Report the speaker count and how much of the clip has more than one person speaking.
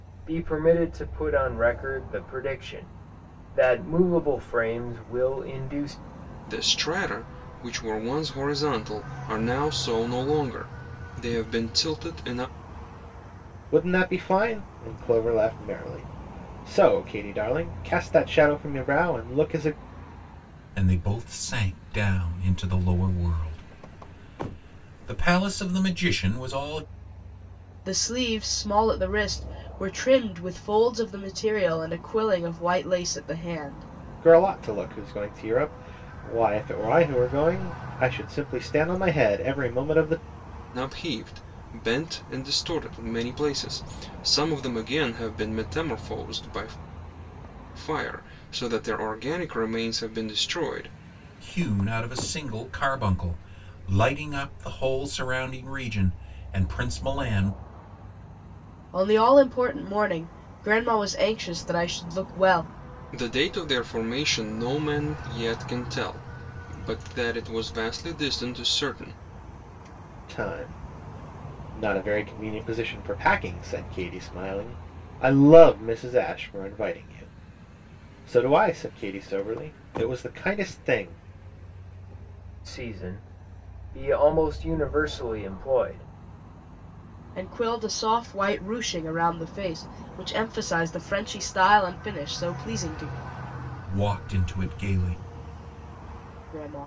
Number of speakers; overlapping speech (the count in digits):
5, no overlap